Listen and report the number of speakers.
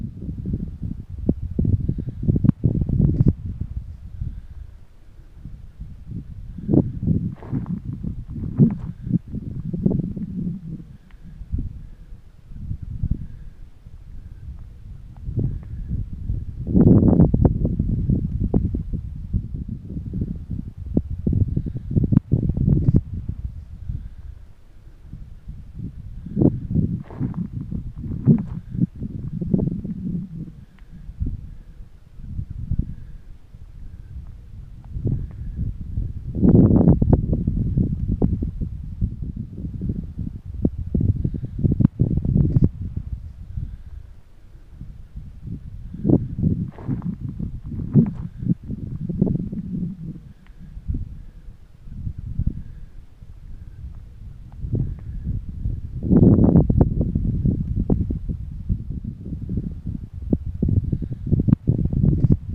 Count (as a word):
zero